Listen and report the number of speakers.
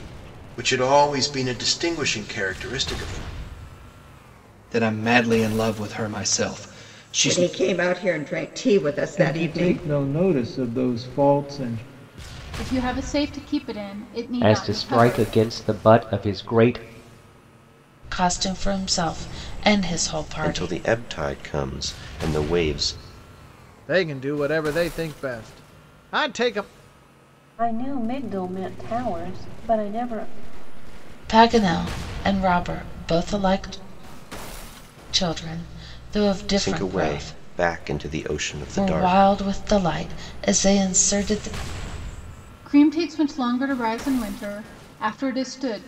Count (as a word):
ten